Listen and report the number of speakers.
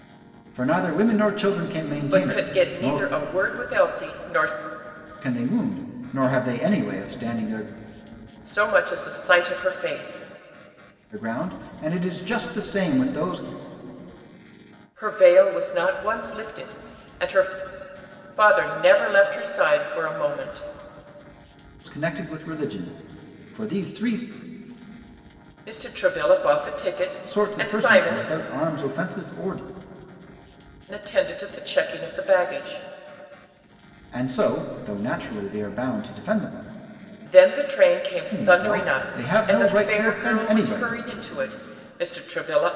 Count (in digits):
2